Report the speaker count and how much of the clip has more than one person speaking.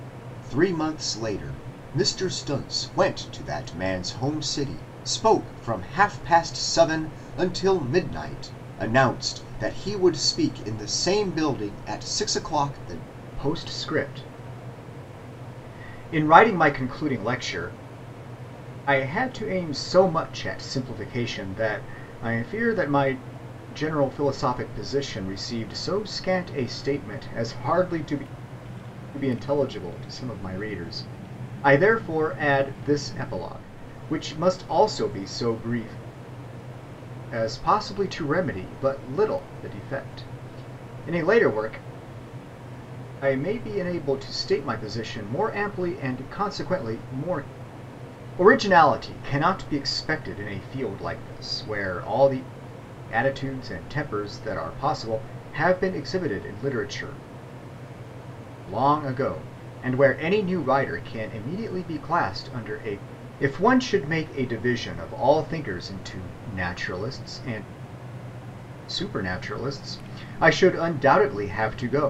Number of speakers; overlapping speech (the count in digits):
1, no overlap